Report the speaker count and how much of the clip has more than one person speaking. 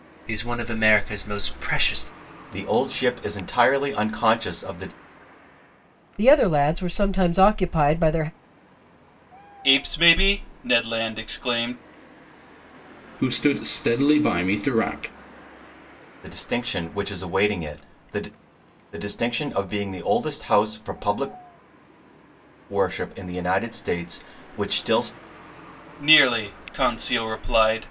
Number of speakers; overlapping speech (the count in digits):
5, no overlap